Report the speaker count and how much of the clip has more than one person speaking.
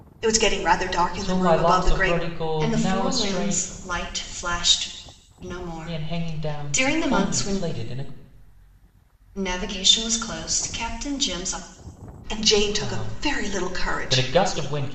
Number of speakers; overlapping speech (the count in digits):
3, about 37%